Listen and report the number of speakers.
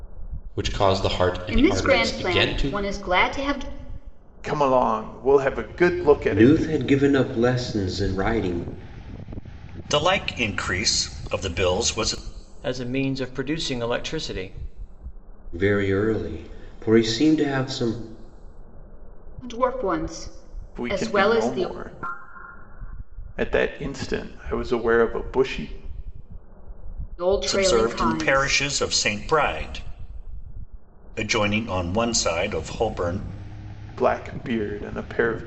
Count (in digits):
6